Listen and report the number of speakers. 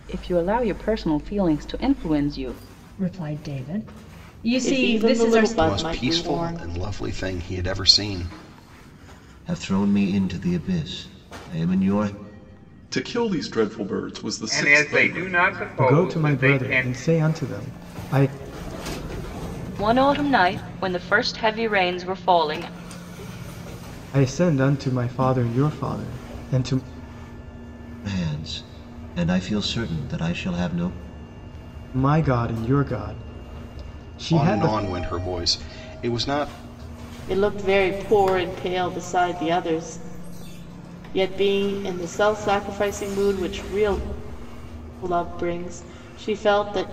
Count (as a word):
nine